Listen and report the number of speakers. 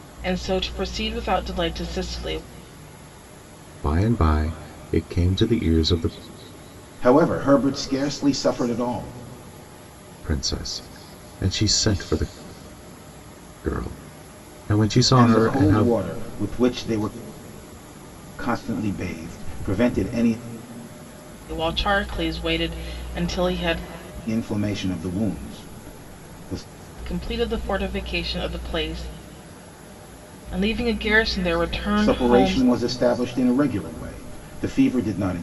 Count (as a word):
three